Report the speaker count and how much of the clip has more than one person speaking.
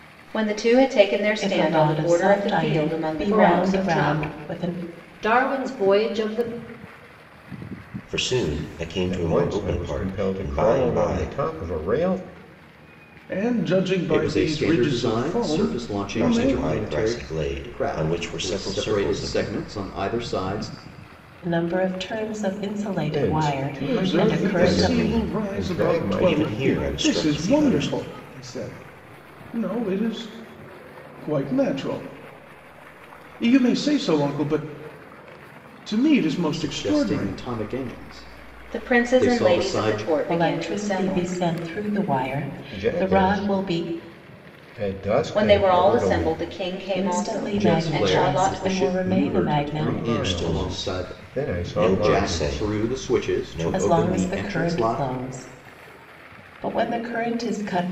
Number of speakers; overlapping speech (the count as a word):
seven, about 50%